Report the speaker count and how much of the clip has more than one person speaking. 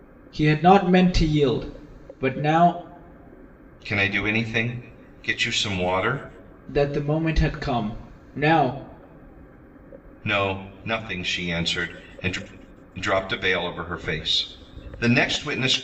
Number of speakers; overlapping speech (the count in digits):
2, no overlap